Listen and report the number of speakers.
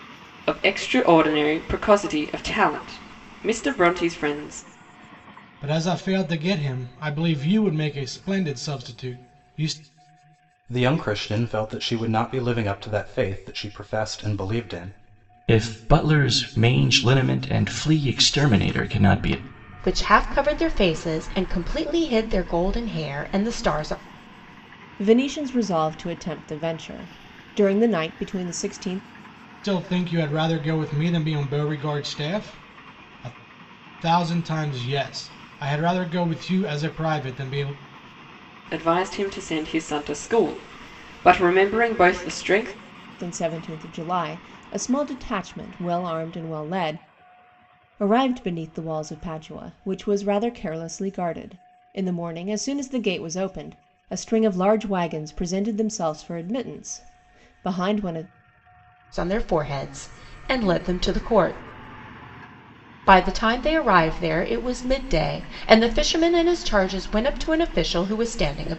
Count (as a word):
six